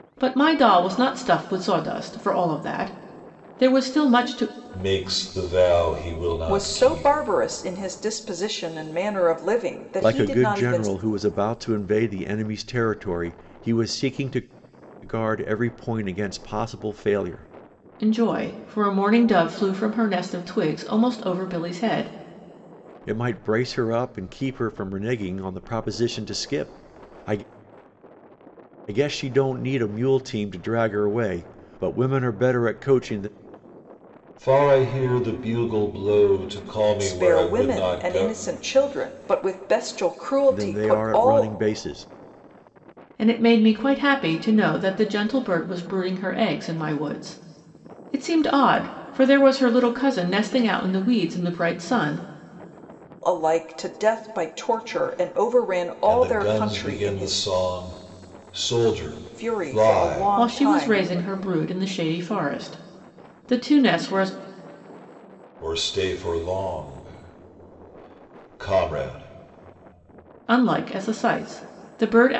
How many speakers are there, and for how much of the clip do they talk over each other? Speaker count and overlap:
four, about 10%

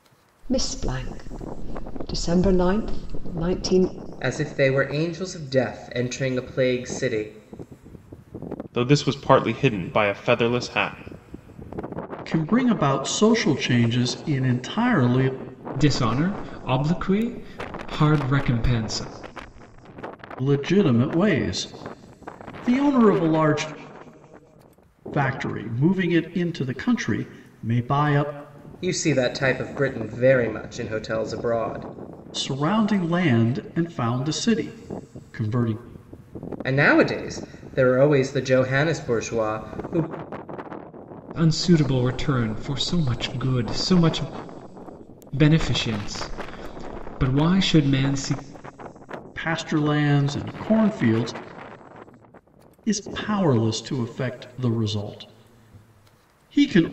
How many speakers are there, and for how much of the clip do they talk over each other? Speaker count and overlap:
five, no overlap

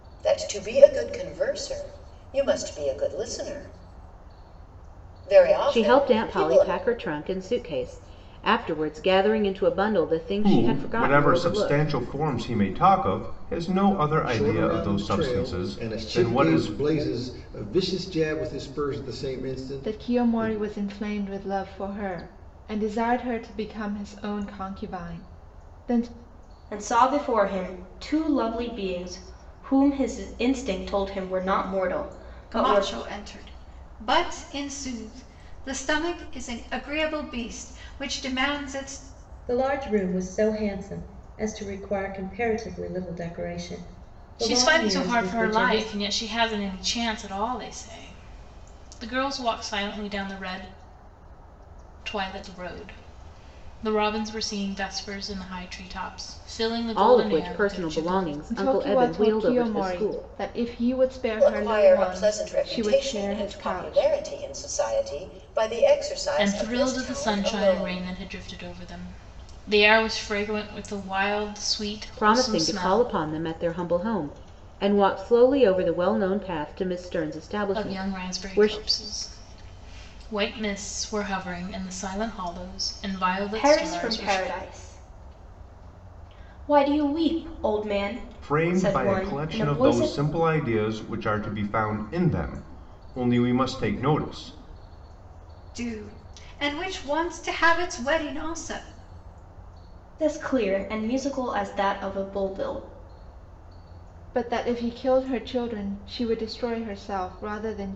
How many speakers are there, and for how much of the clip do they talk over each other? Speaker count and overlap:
nine, about 19%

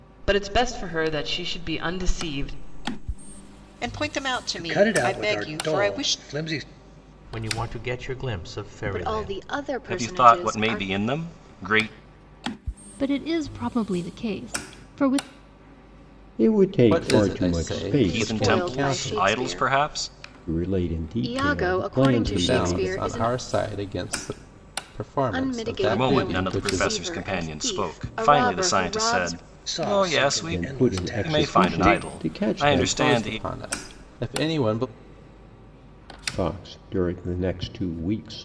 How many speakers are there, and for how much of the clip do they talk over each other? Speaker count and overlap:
nine, about 43%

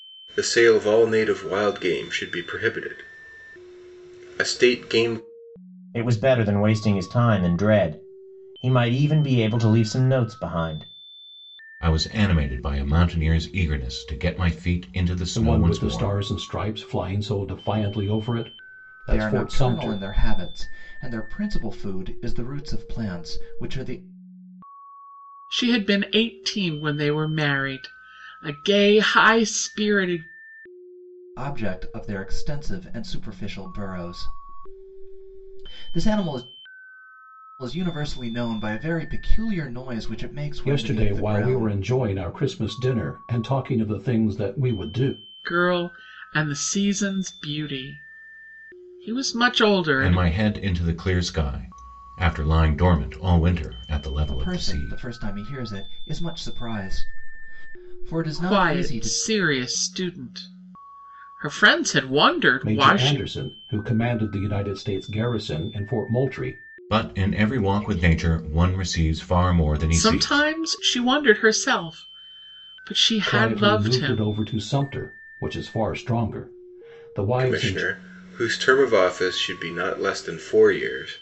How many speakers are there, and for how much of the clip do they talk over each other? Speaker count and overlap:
six, about 10%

